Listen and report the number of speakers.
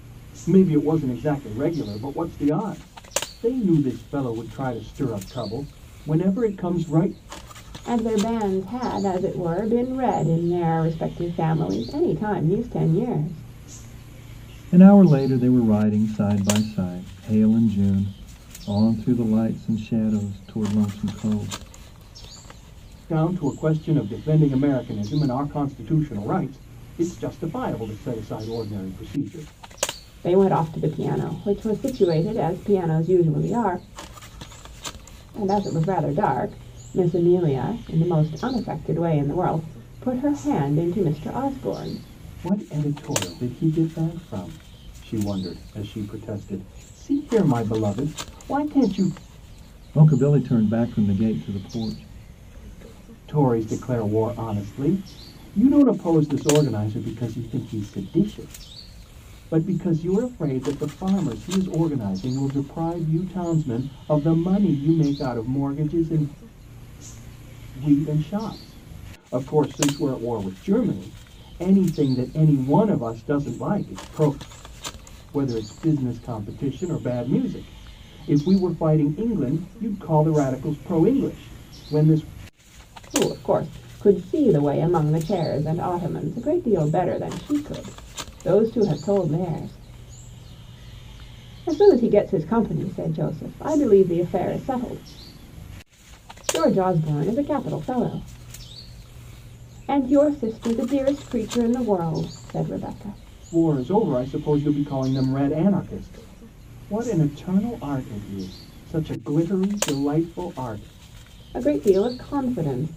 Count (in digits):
3